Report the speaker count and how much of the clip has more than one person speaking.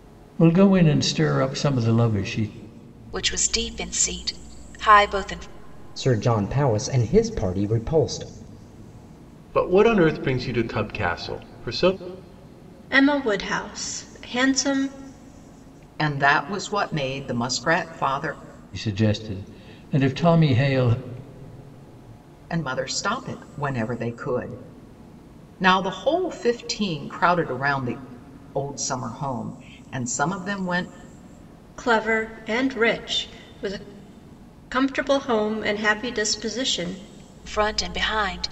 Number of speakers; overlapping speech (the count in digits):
6, no overlap